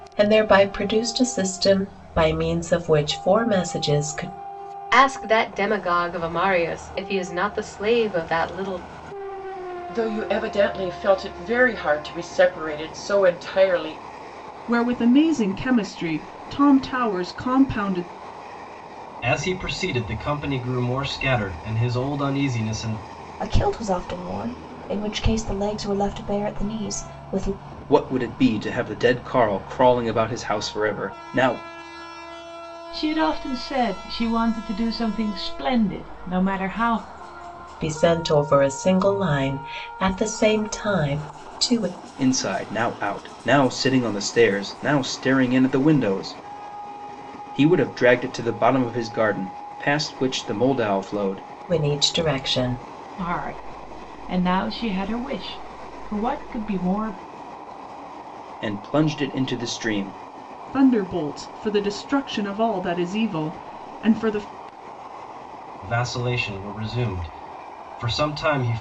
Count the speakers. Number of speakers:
8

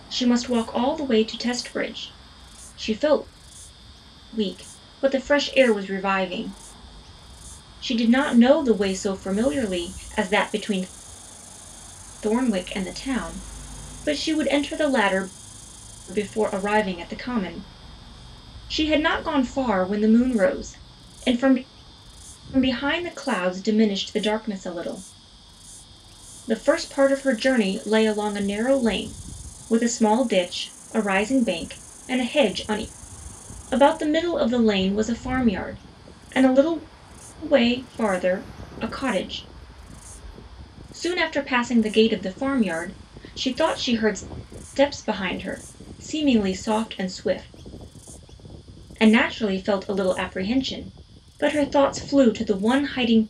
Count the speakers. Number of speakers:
1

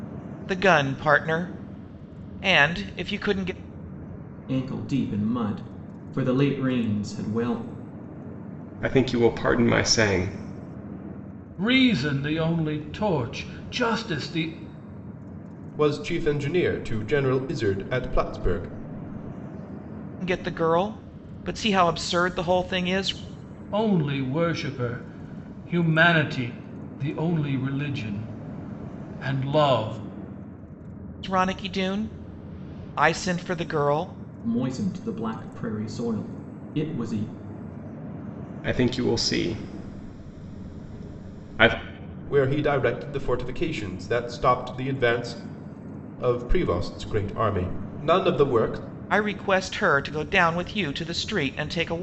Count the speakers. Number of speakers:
5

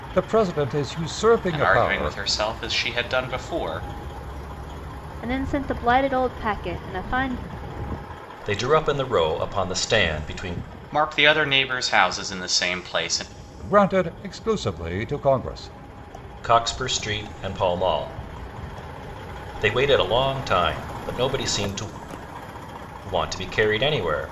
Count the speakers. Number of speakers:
4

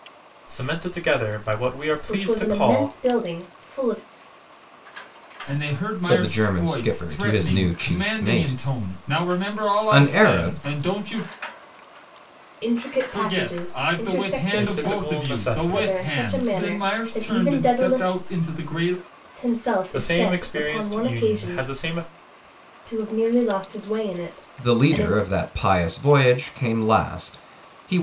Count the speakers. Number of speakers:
4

